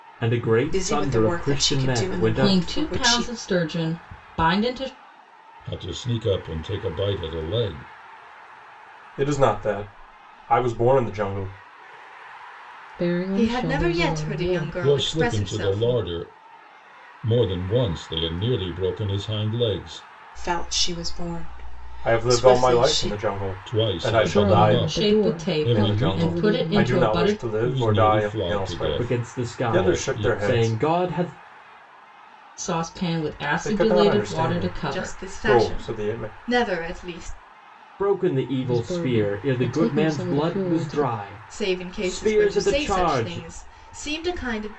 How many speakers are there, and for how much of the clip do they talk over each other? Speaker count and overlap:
seven, about 46%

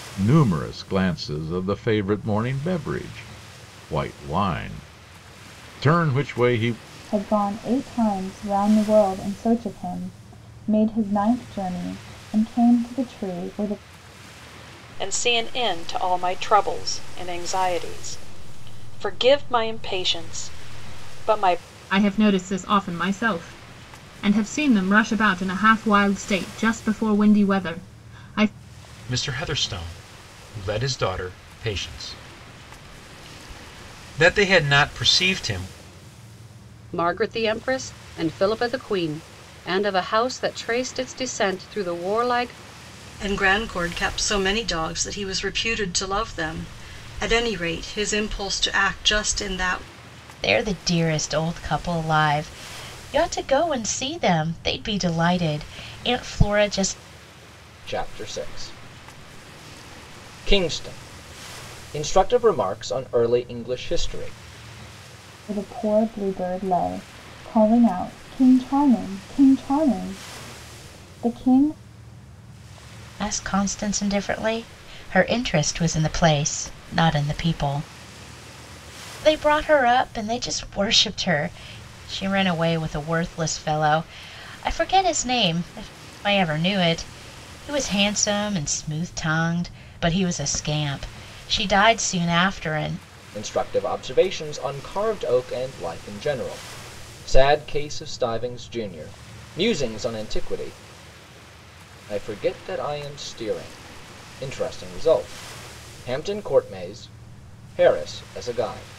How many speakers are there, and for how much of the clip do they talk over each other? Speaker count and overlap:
nine, no overlap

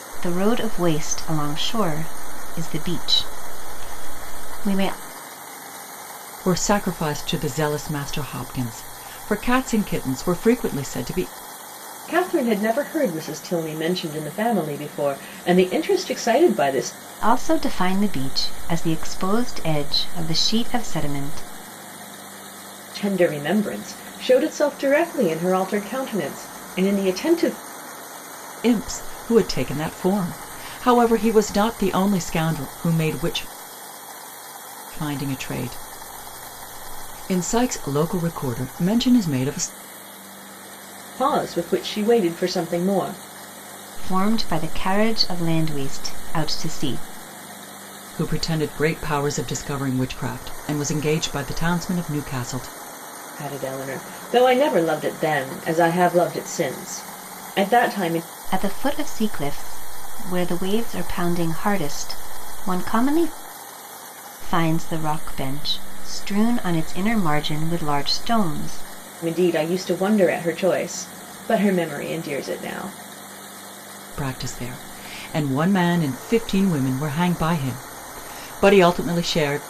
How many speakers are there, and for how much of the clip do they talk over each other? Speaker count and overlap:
three, no overlap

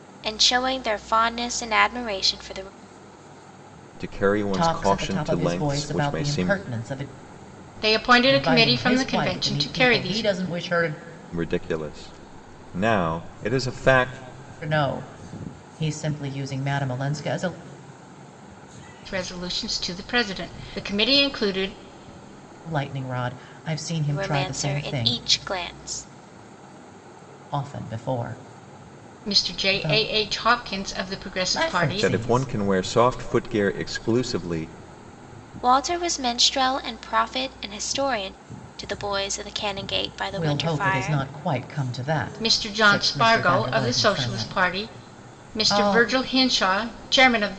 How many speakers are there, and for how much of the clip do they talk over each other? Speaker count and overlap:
four, about 23%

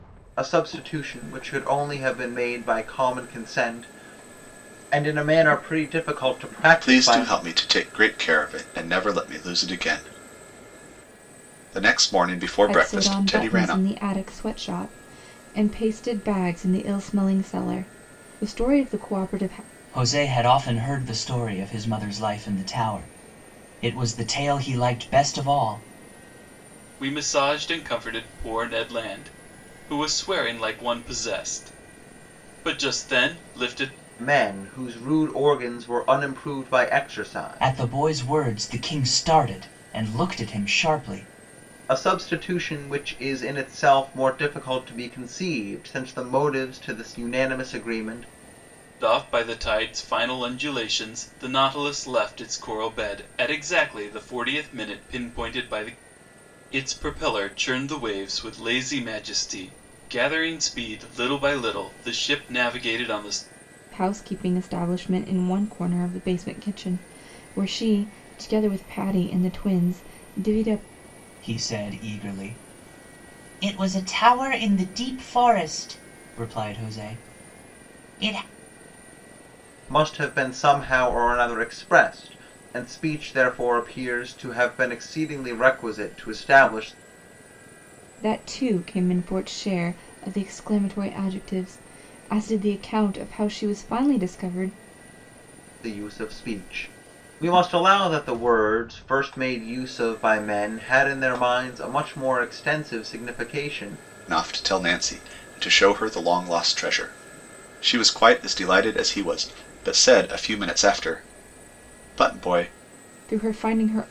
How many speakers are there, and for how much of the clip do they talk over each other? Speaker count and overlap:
five, about 2%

